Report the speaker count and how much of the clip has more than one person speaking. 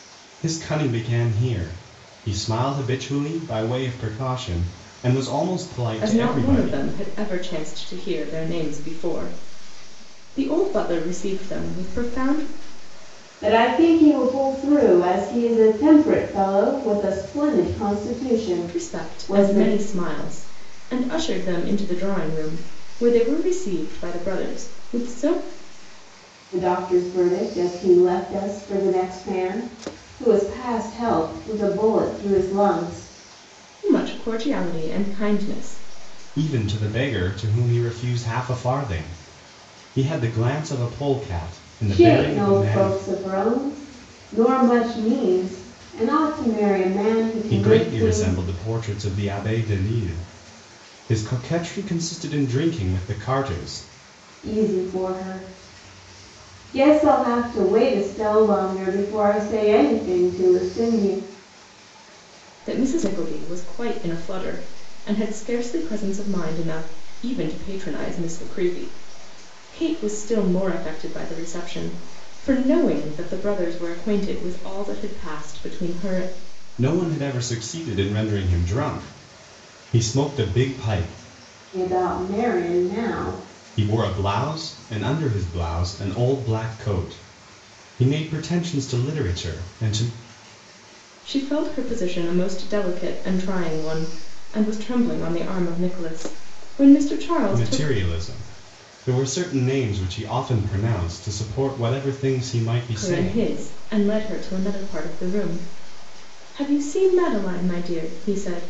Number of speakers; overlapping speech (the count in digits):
3, about 5%